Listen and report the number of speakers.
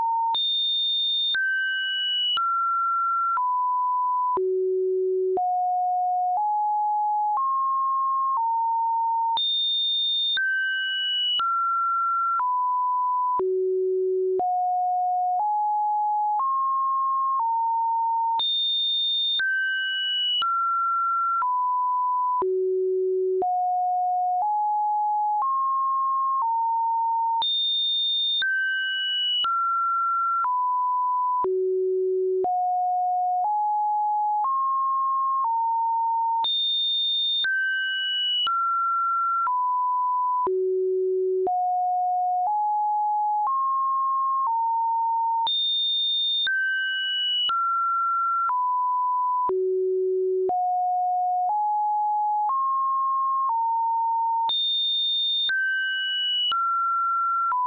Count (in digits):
0